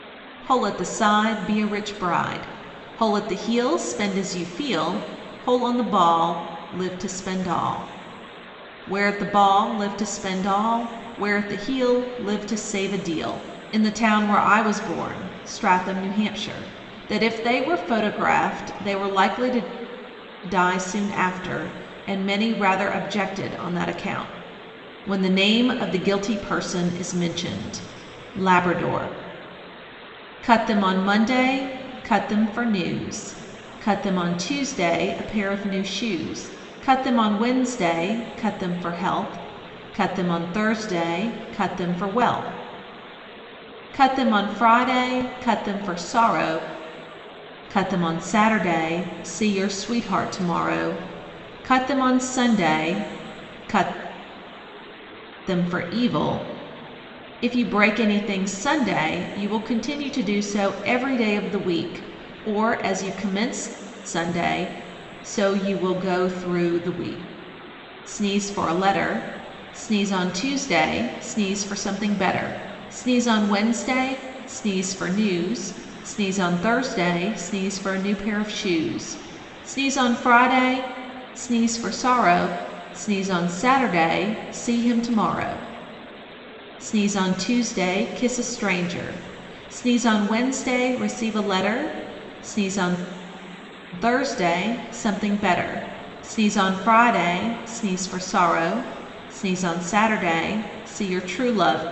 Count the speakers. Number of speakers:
one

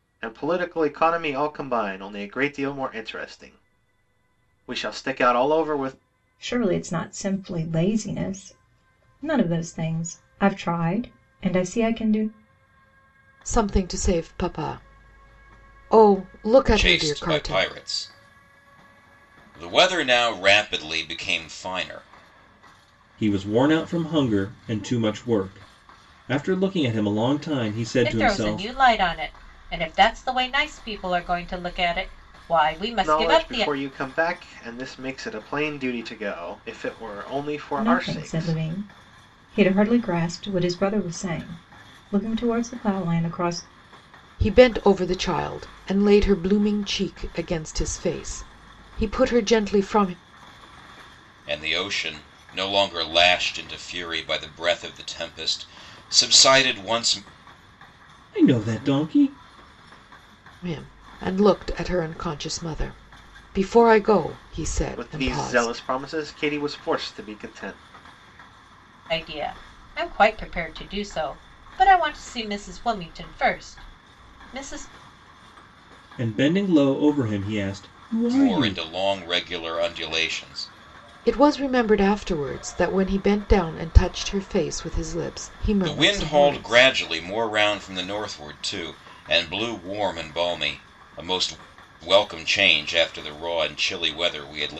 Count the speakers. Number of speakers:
six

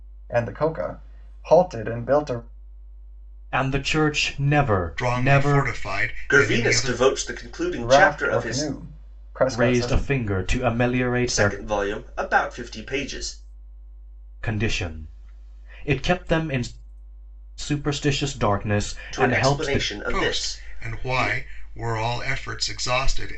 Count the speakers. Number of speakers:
four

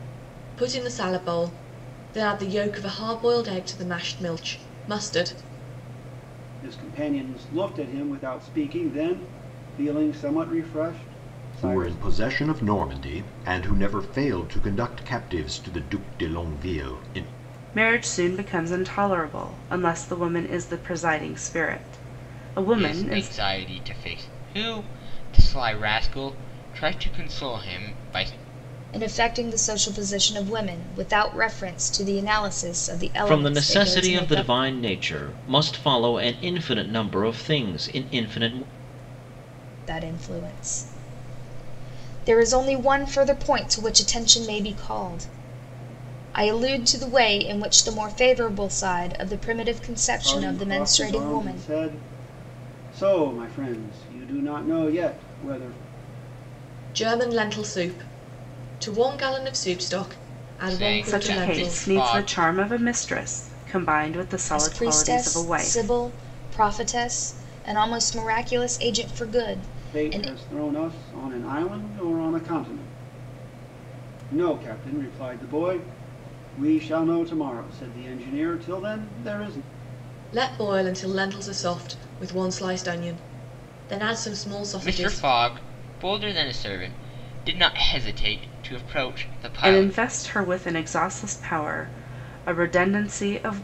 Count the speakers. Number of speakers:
seven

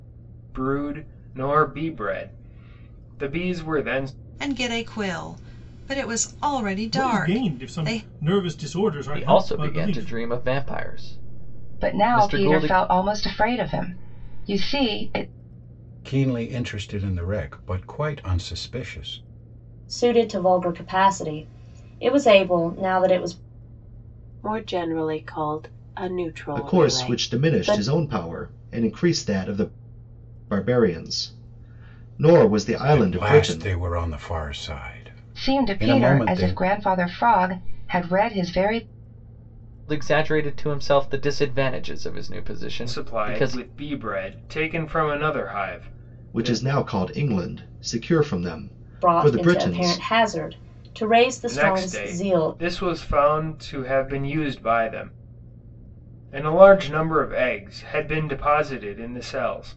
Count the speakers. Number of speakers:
nine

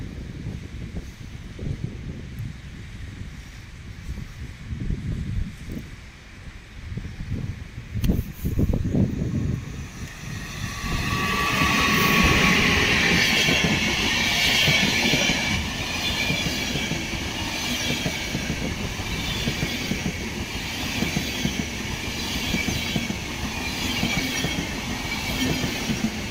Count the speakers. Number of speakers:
zero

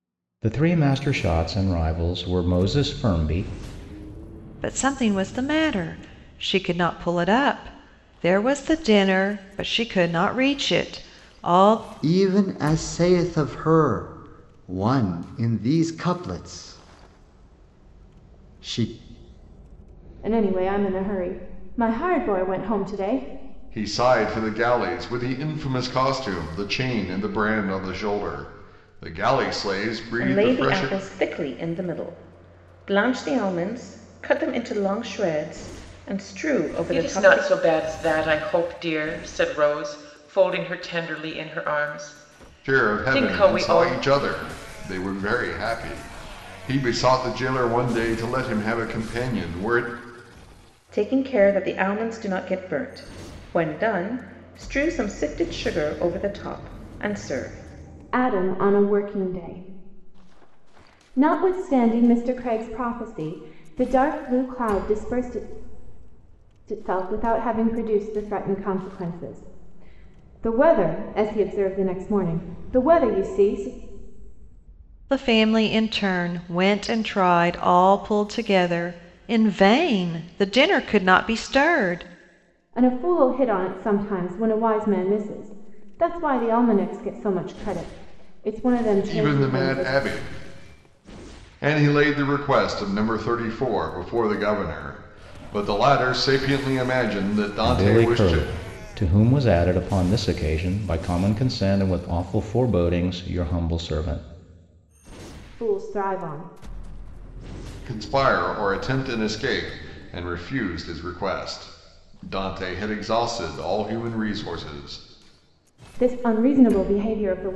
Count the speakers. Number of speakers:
seven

